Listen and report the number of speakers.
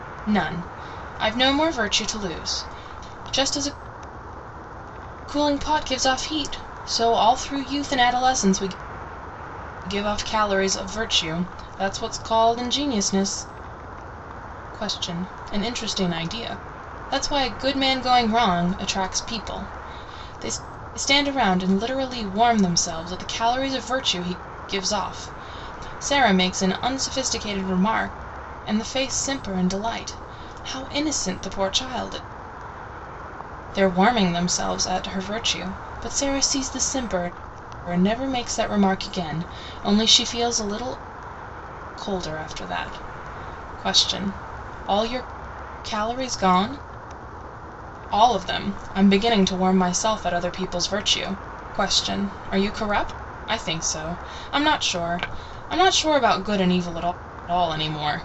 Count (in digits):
1